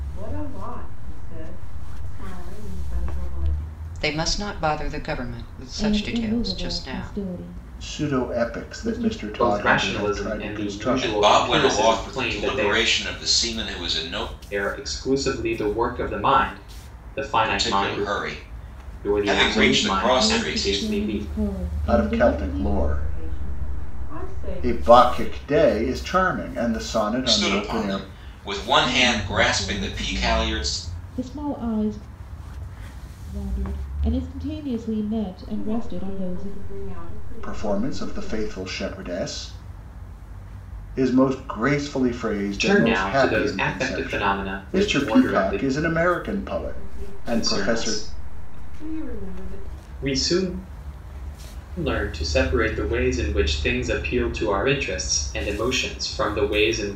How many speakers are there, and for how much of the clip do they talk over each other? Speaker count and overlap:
6, about 42%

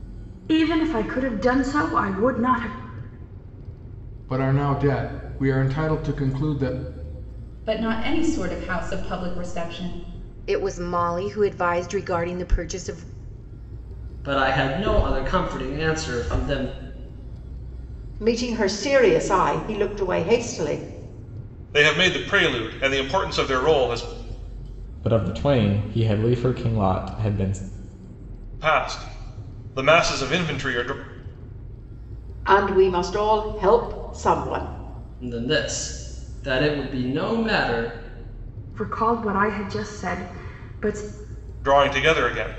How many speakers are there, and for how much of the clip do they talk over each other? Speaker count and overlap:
8, no overlap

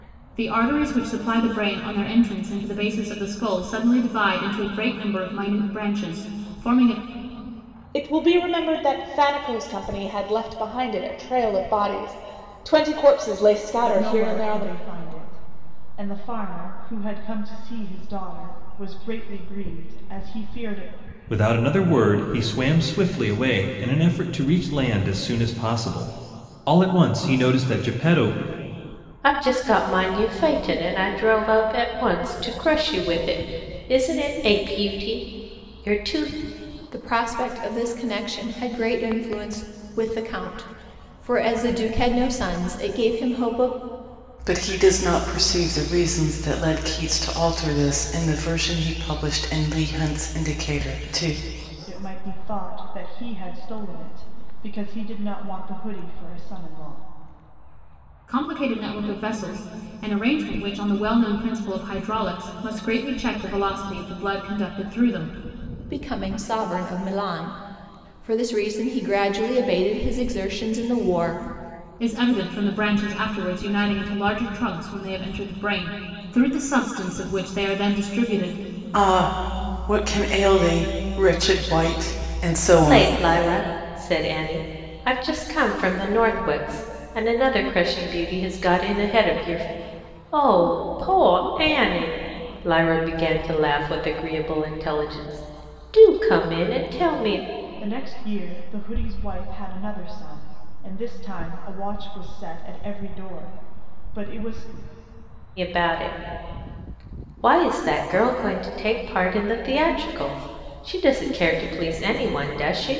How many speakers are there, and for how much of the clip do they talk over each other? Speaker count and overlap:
7, about 1%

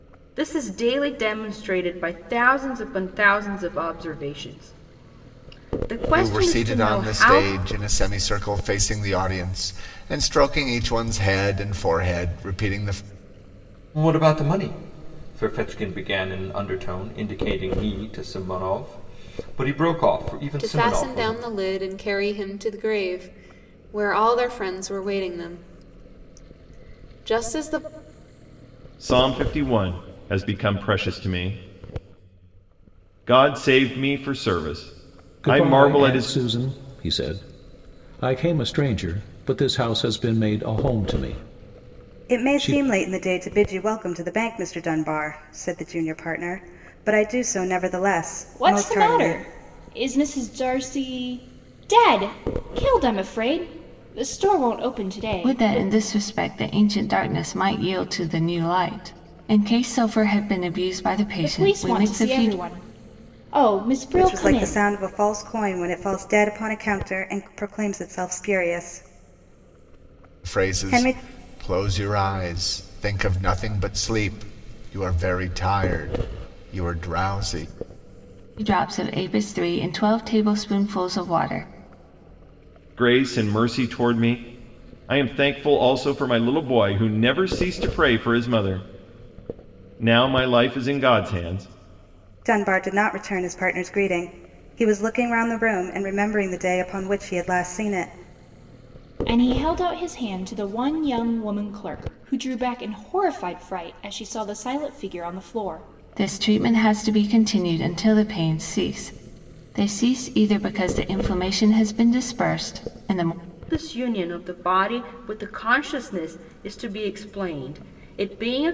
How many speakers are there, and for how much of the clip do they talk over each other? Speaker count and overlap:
9, about 7%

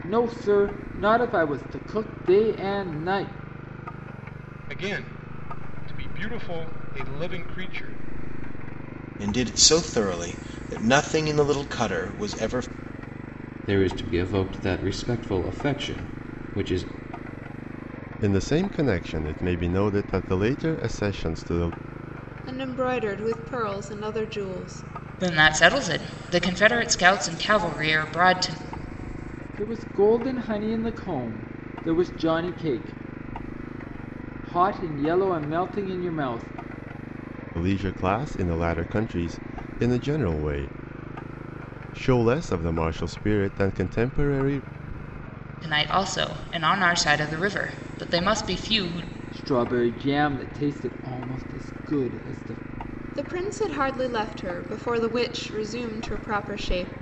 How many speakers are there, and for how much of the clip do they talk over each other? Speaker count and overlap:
7, no overlap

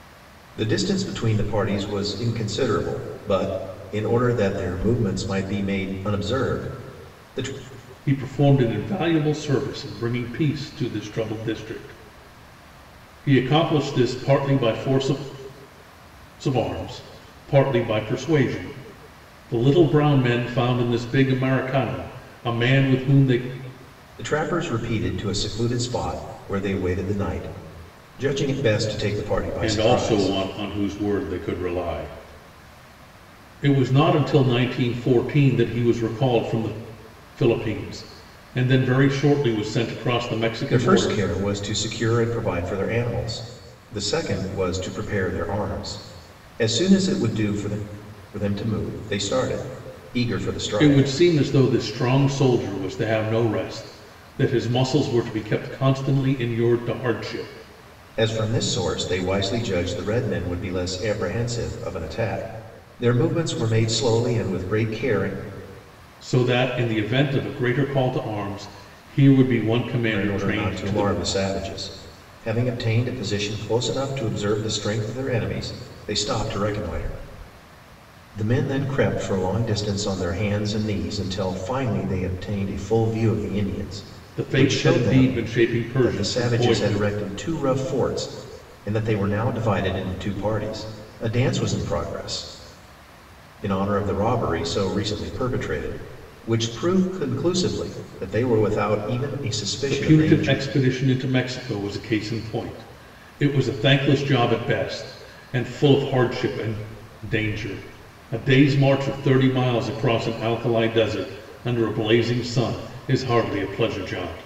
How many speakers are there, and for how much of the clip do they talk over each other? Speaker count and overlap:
2, about 5%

